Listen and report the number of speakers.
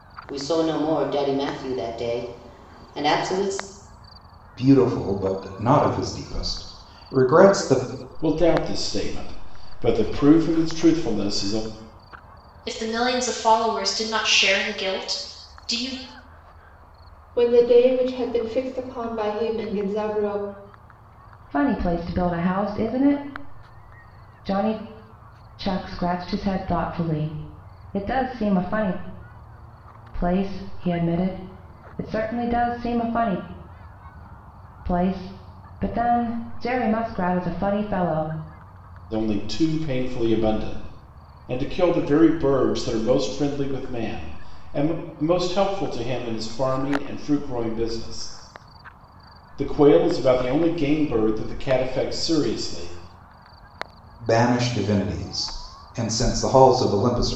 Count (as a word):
six